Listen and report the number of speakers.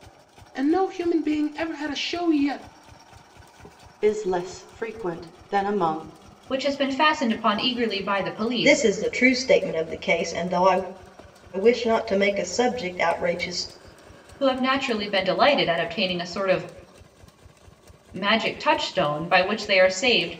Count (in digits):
4